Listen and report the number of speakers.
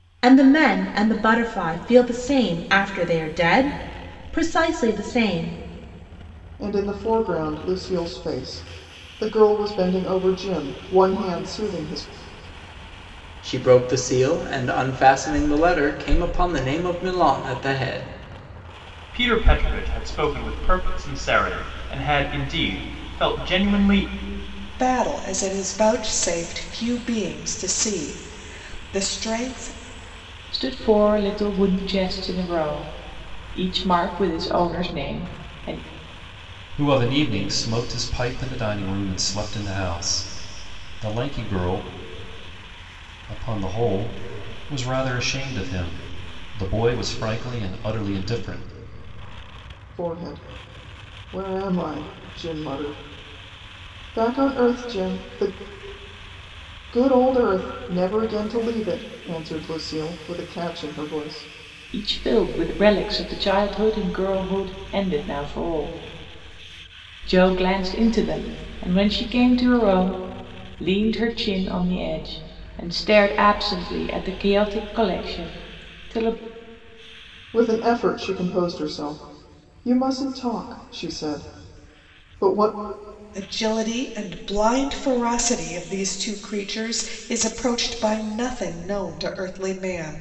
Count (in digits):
7